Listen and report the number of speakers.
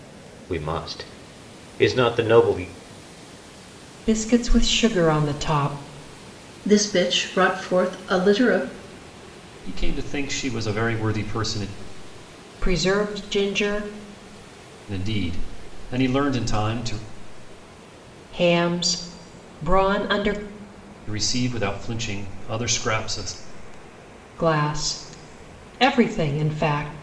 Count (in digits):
4